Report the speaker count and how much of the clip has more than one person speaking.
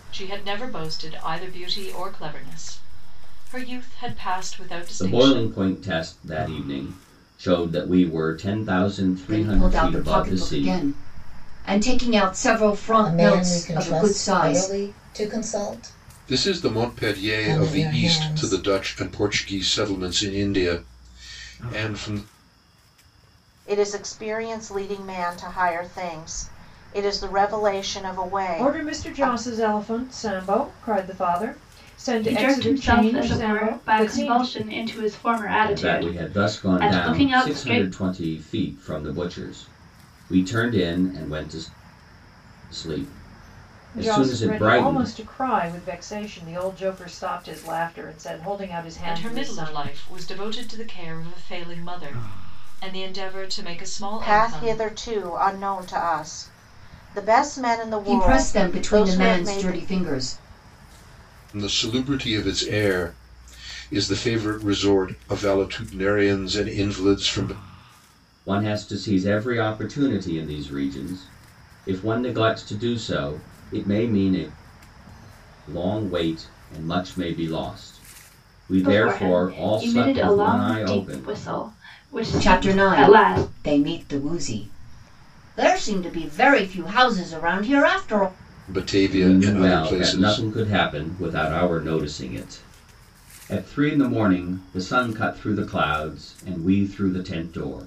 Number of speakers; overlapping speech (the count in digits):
8, about 22%